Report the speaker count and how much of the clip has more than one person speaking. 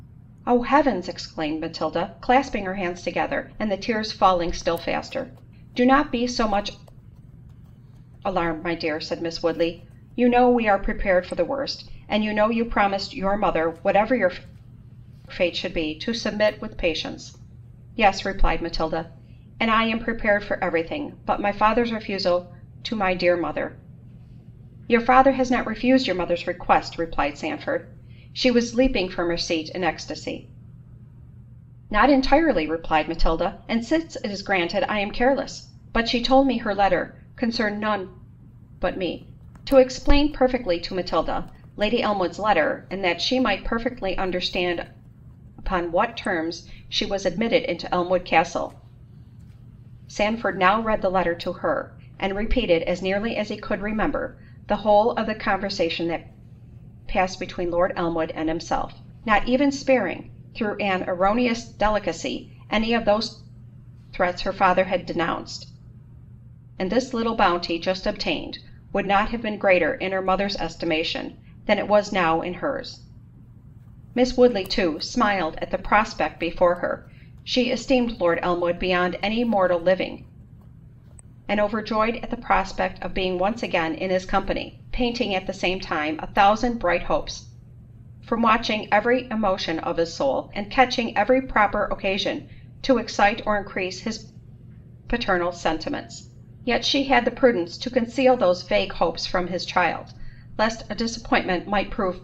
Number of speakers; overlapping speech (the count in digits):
1, no overlap